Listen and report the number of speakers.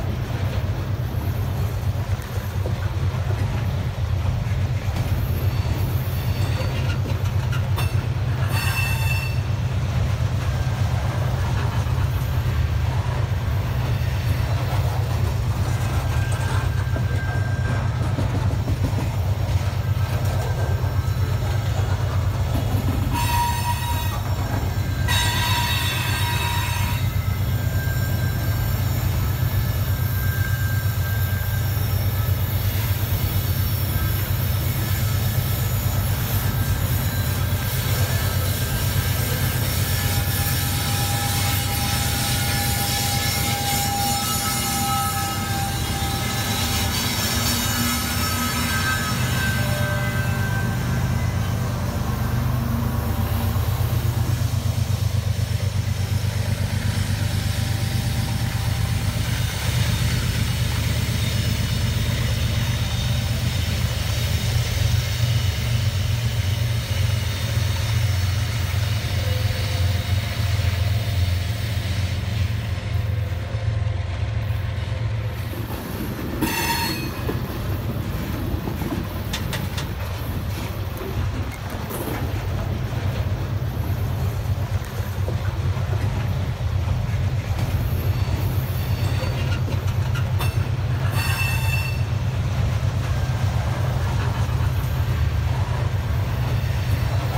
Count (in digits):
0